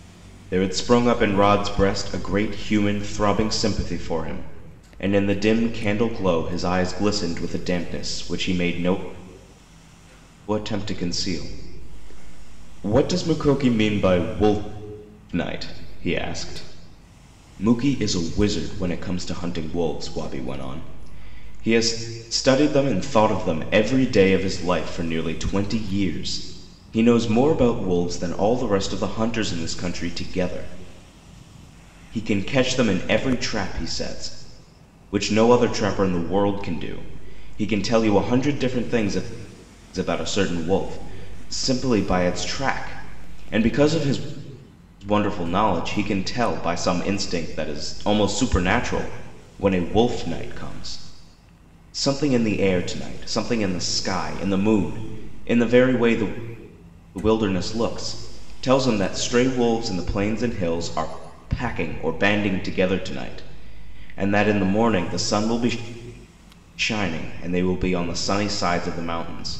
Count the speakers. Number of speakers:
1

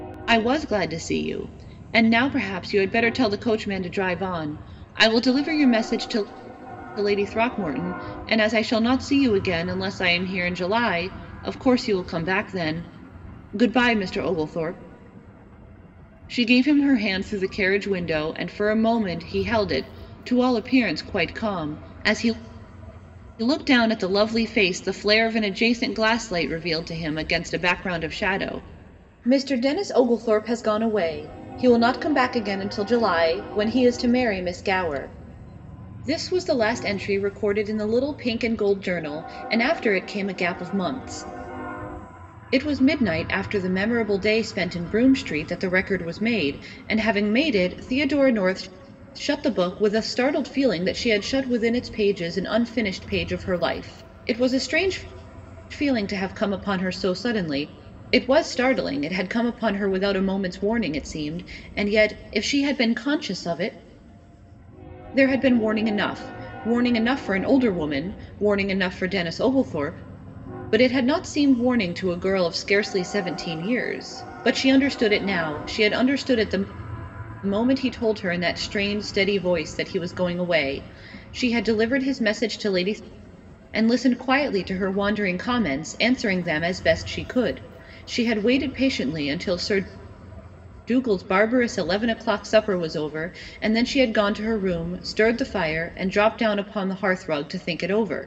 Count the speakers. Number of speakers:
1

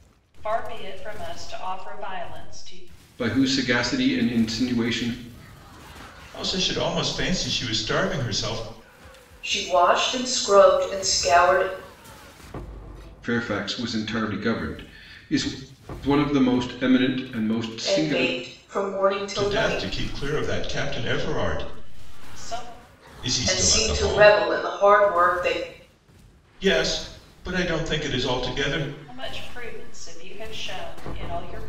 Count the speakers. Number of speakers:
4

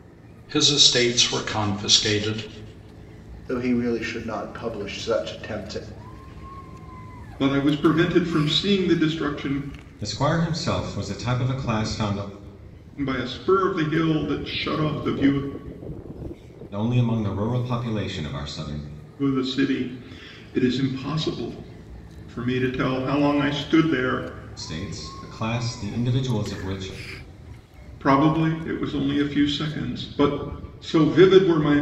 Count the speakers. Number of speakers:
4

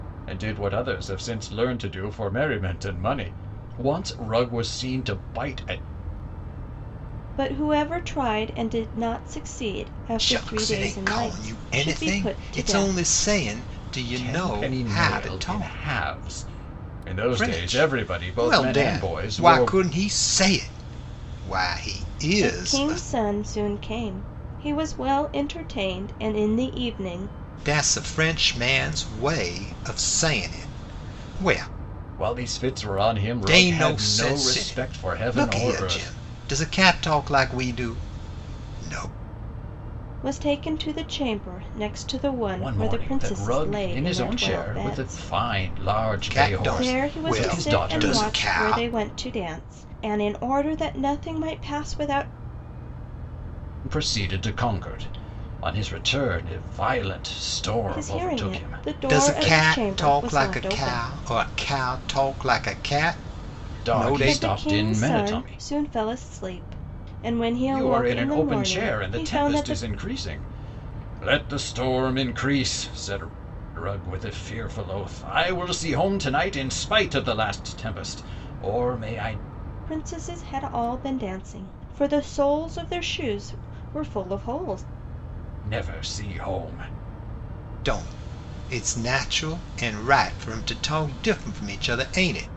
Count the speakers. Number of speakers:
3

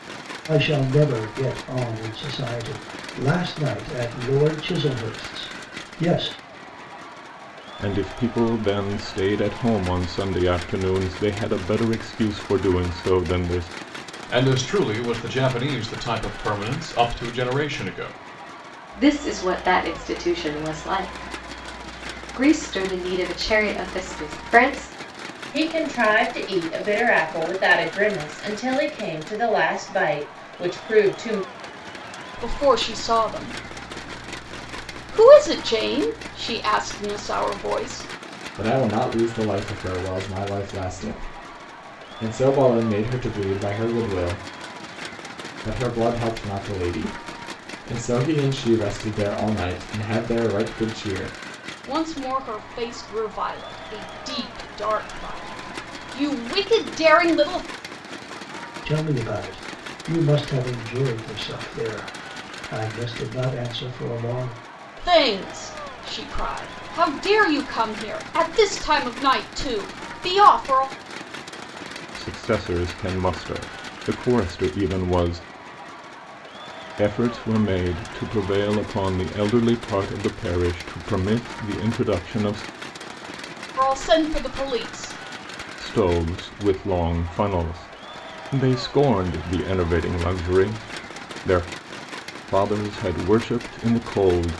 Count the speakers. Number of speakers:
7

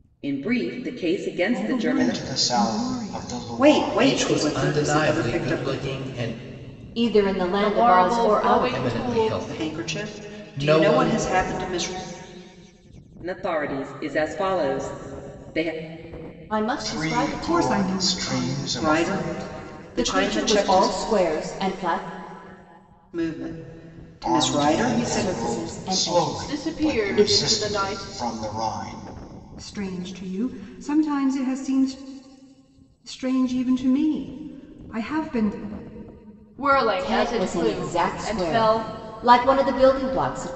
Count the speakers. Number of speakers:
7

